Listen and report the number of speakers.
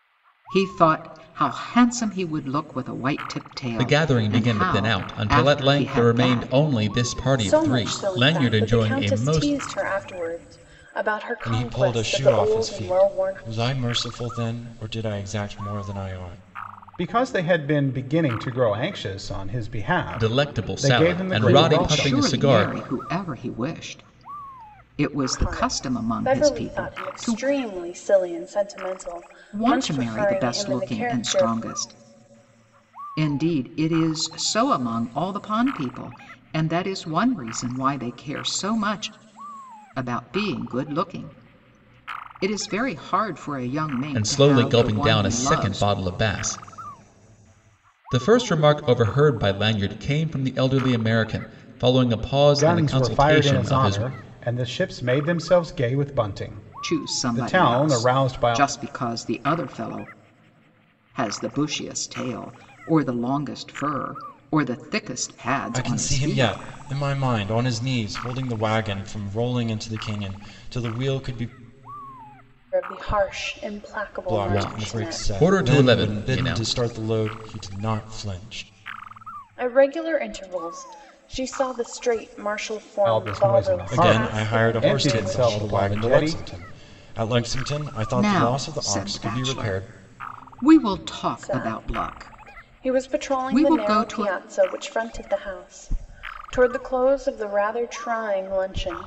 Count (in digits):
5